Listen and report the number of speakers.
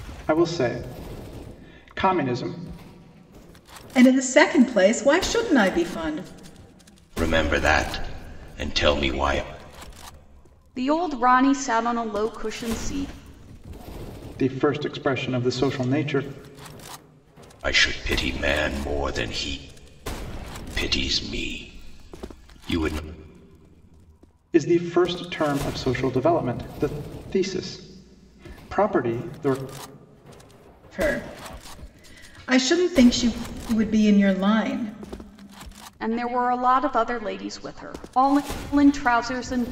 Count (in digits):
4